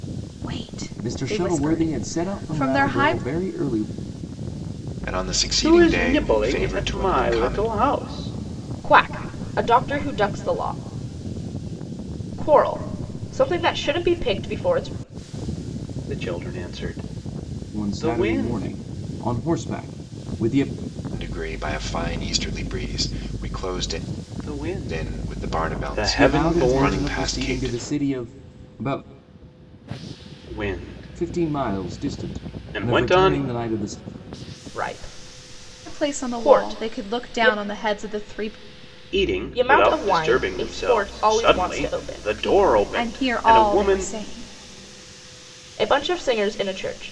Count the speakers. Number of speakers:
five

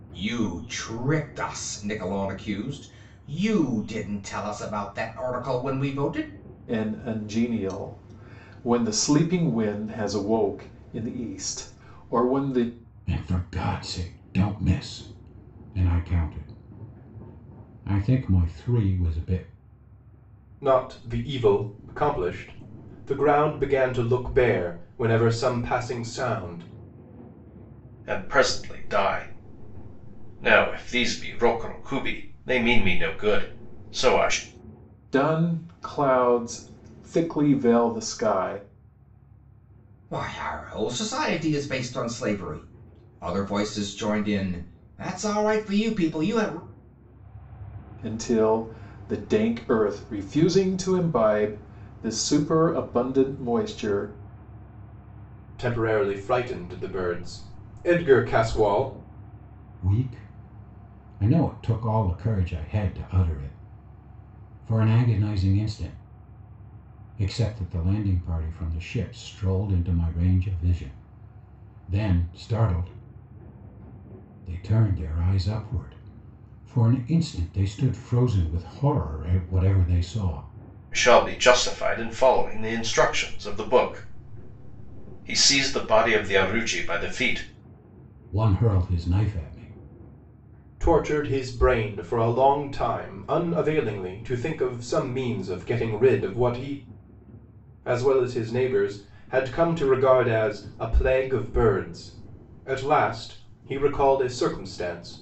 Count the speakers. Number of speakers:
five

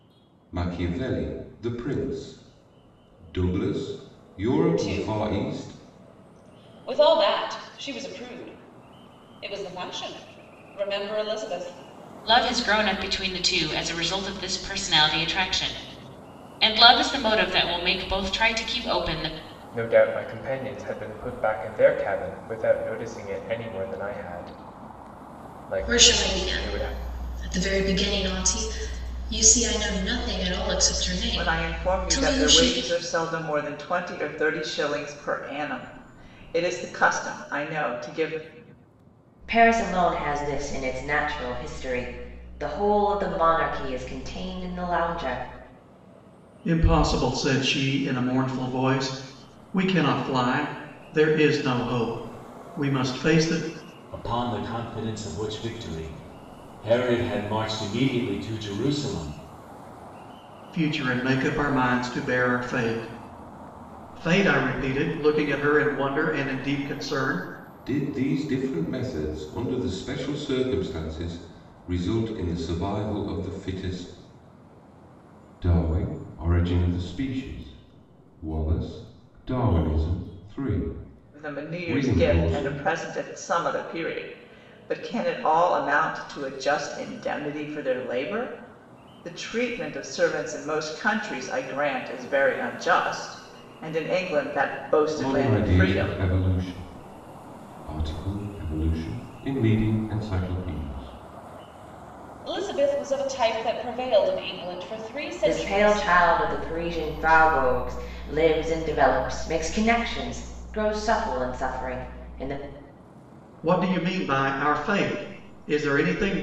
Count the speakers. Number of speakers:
nine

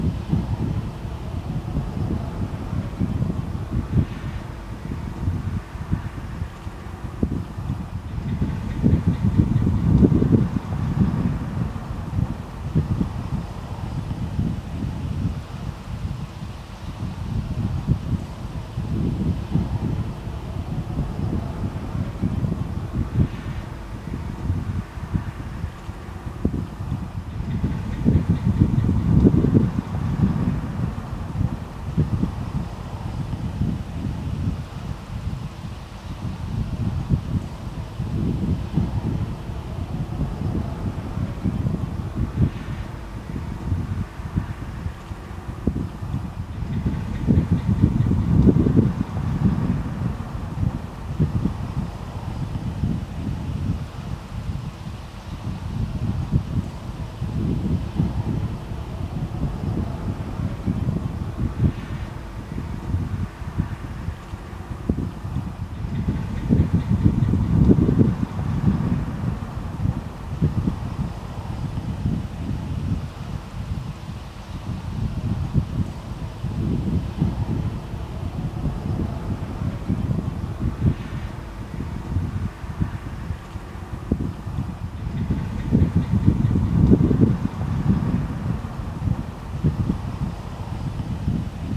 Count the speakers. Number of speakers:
zero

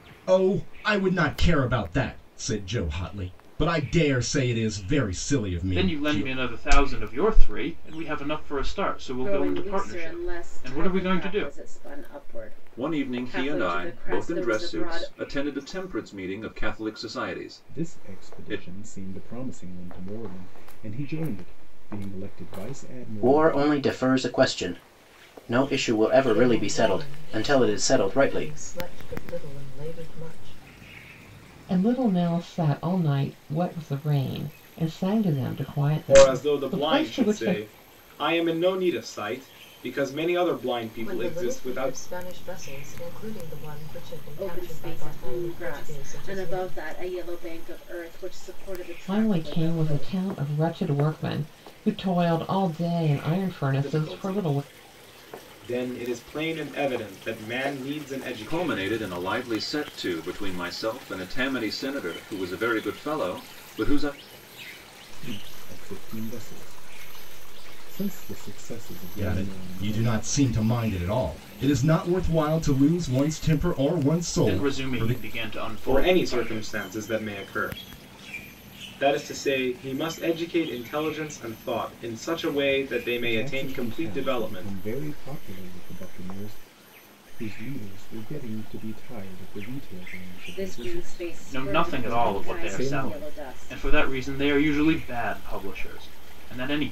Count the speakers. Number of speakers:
nine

